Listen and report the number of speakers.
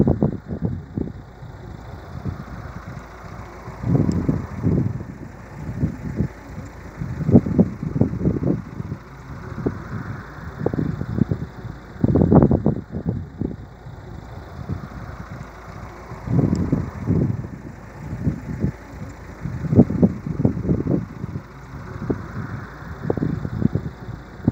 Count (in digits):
0